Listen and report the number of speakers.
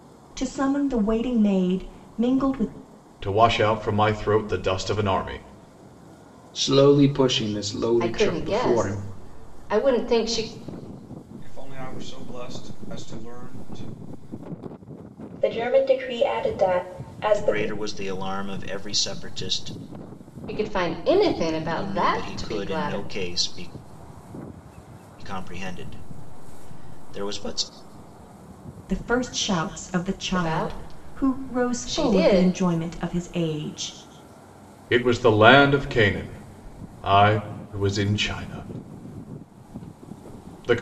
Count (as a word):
seven